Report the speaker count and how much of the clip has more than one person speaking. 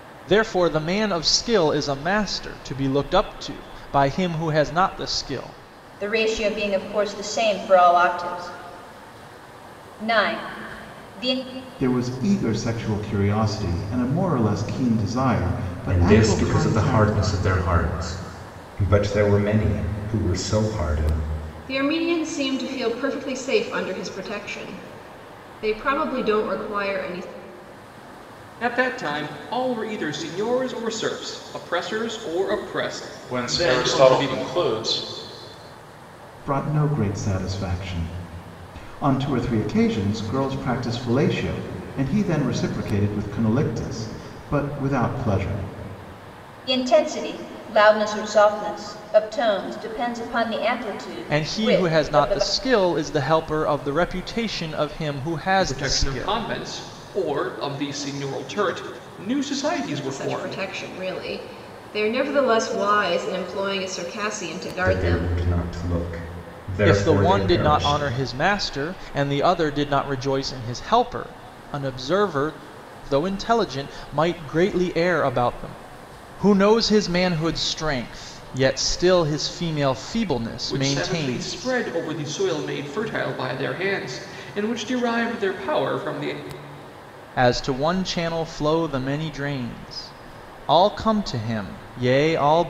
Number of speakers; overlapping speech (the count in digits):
7, about 9%